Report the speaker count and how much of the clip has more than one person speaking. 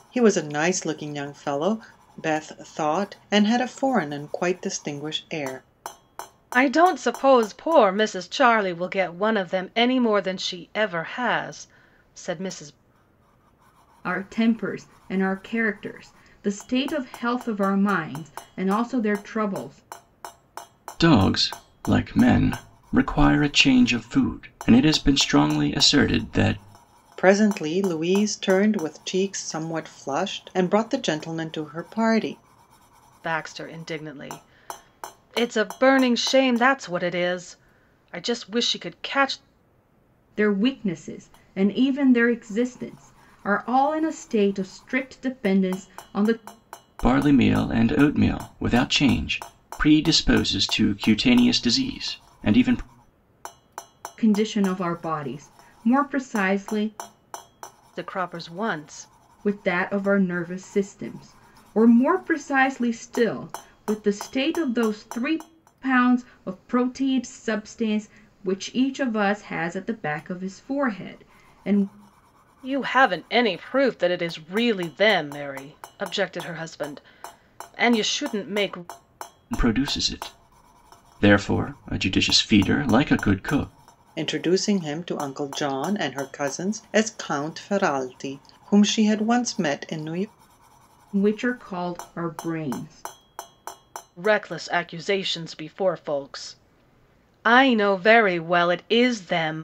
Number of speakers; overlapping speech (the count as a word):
four, no overlap